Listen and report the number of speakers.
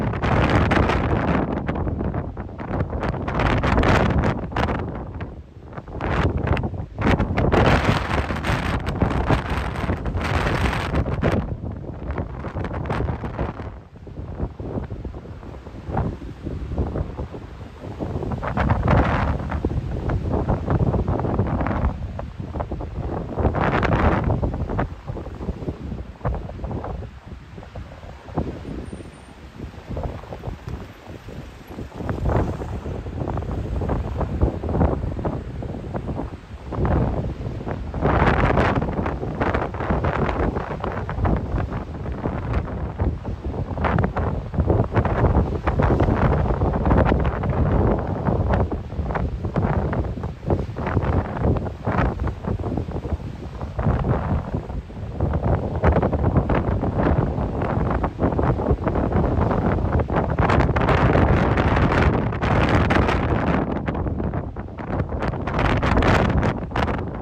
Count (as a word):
zero